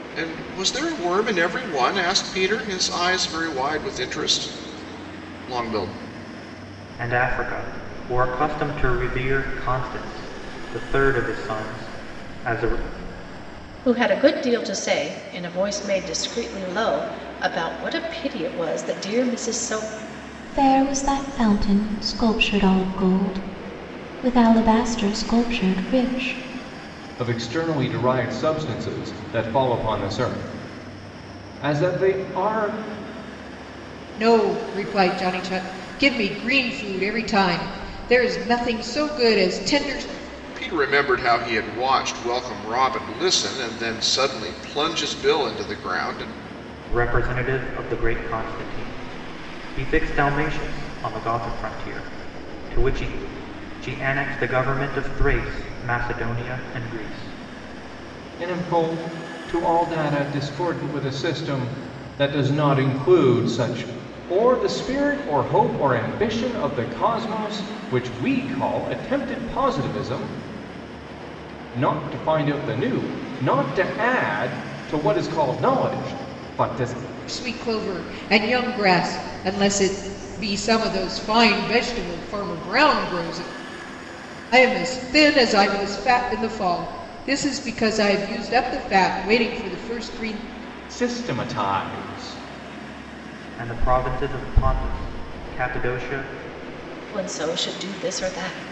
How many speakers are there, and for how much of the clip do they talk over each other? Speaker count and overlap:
six, no overlap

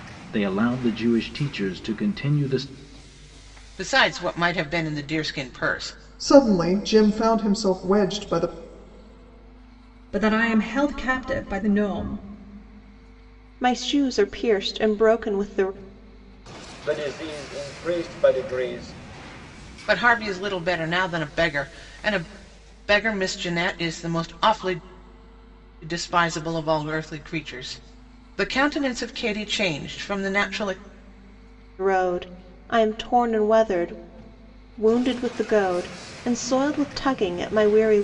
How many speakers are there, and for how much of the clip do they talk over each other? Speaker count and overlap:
six, no overlap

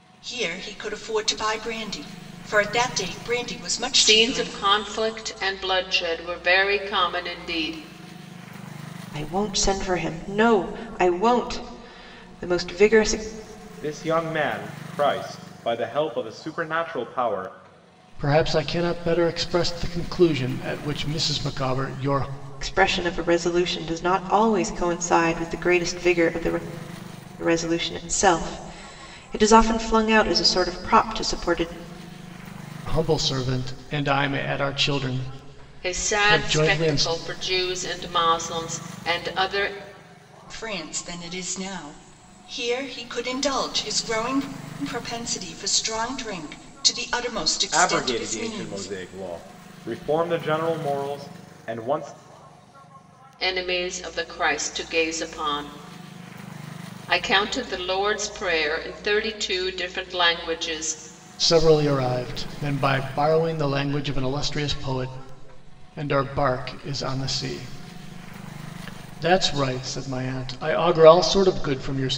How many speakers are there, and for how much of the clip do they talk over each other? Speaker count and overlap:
five, about 4%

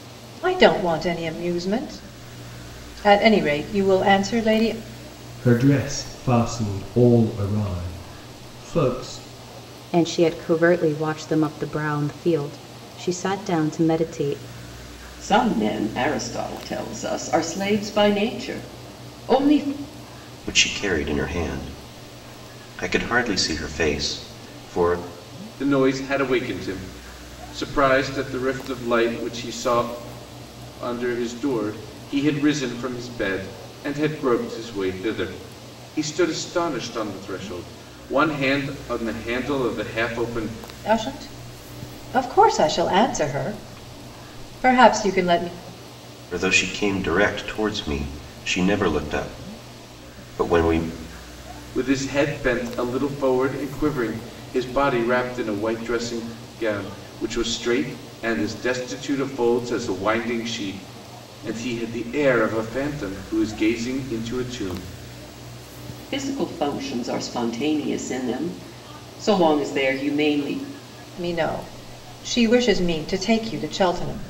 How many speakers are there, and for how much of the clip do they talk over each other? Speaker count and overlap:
six, no overlap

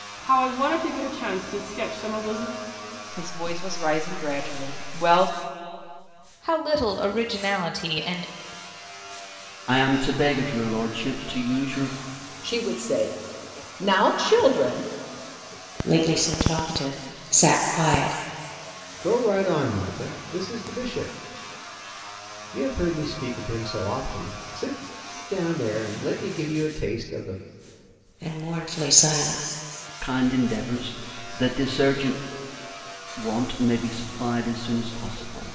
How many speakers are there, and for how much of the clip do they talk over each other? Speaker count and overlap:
seven, no overlap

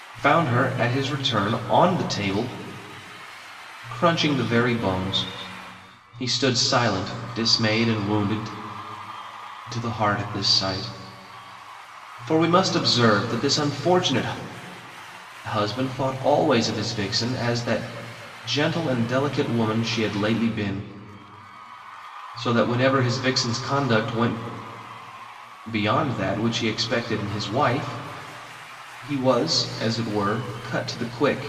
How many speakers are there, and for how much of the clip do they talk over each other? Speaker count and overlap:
one, no overlap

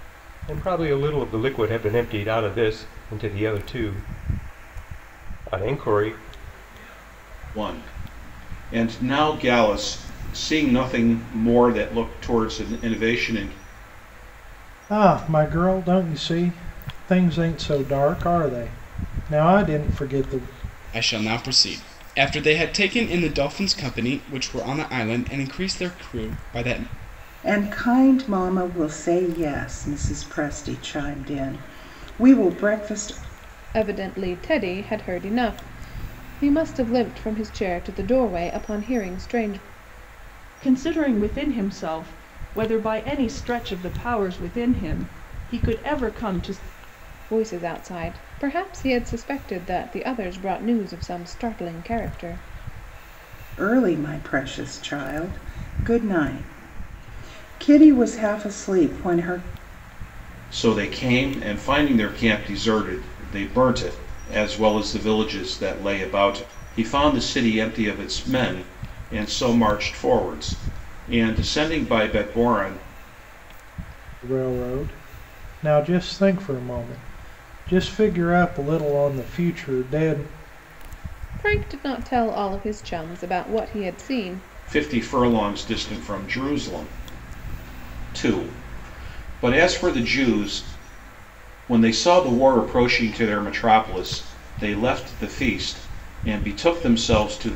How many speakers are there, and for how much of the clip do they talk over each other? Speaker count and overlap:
seven, no overlap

